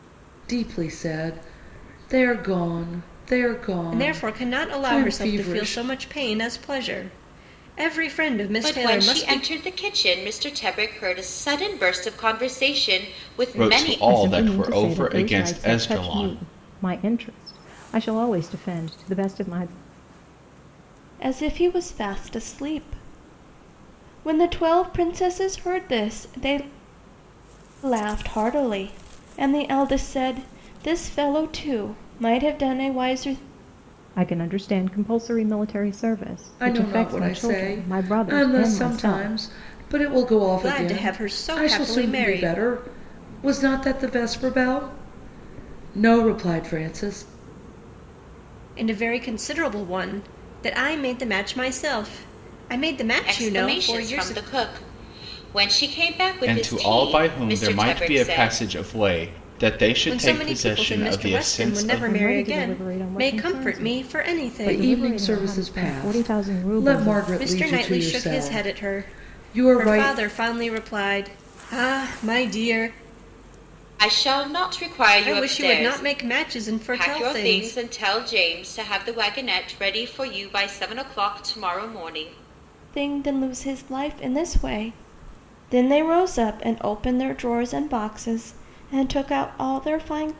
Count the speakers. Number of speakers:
six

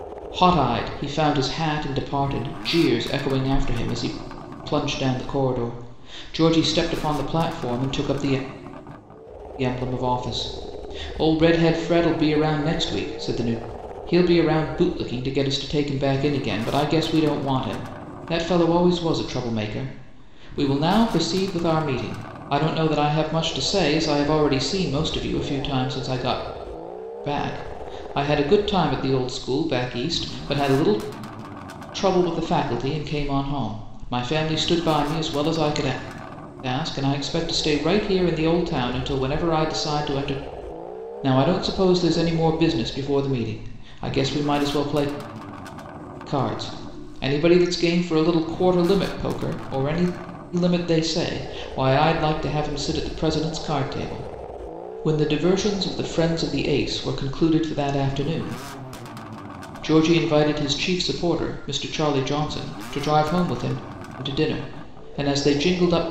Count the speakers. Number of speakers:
one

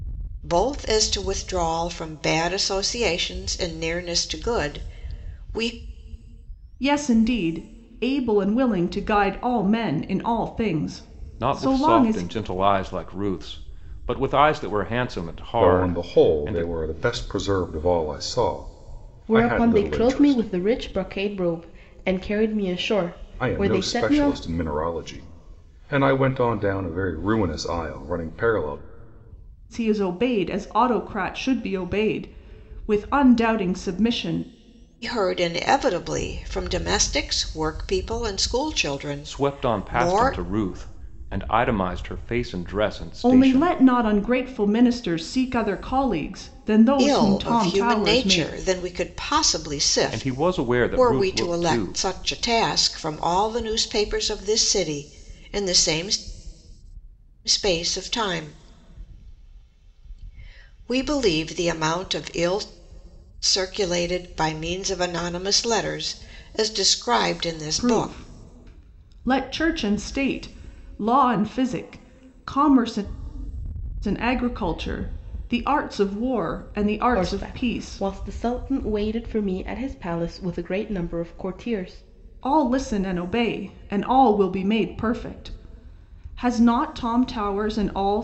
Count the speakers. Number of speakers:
five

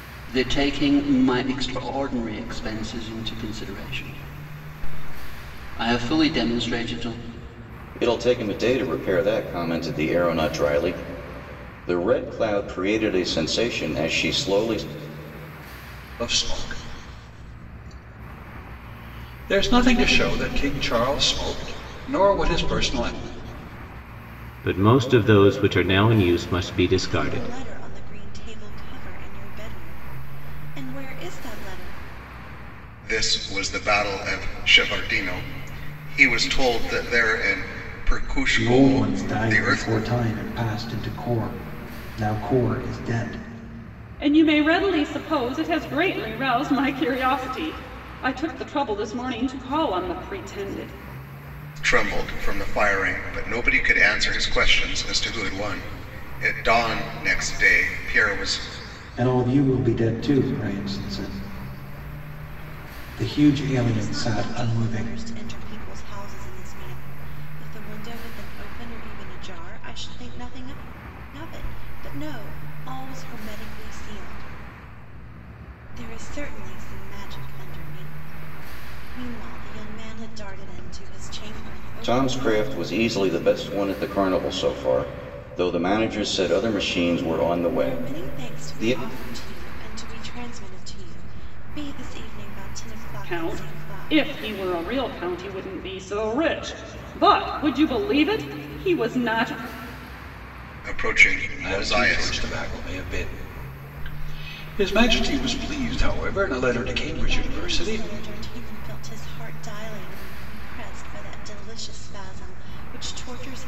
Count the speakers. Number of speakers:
eight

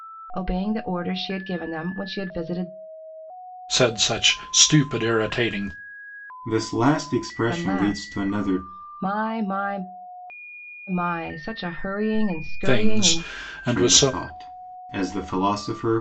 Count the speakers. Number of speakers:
three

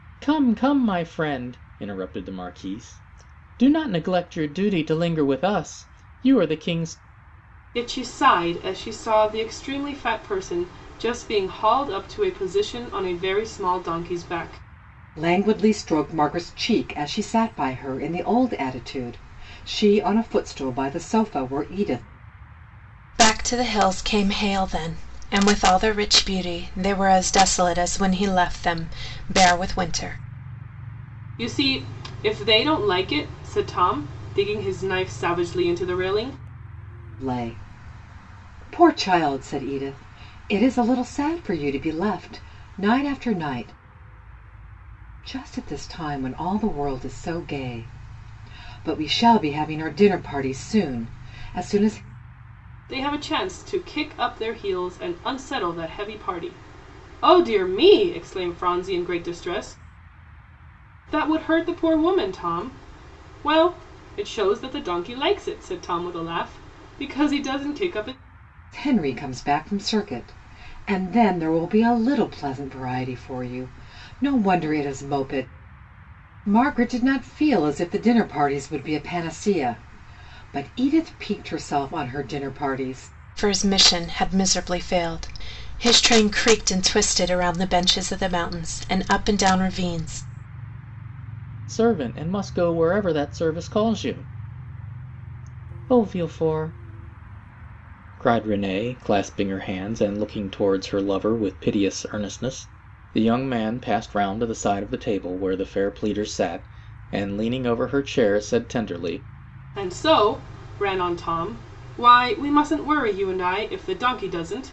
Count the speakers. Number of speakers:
four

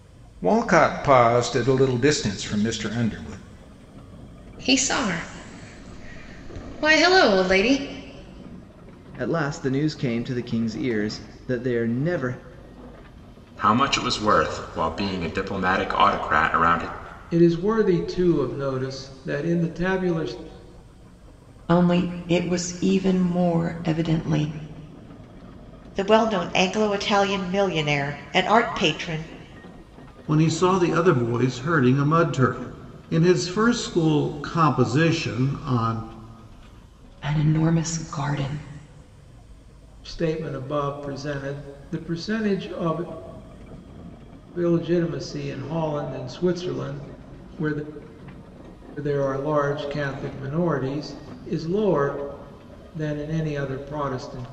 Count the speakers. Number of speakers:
eight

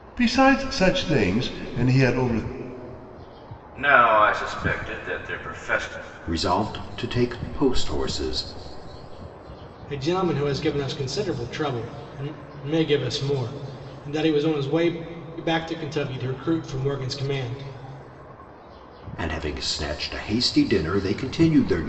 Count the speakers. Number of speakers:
four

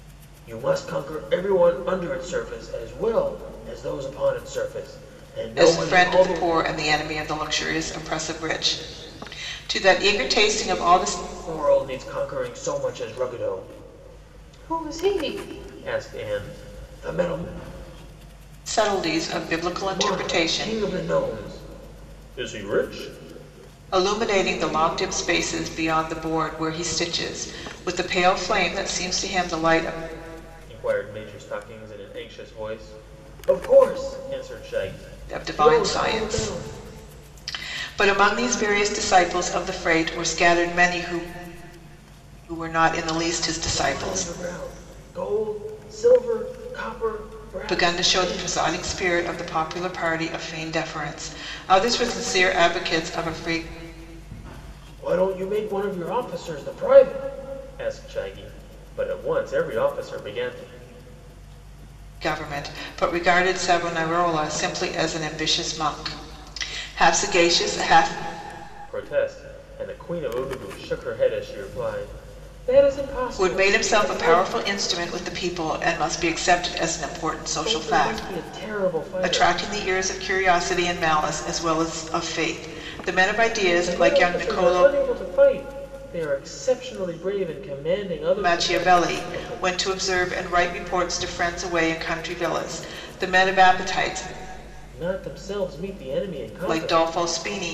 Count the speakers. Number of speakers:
two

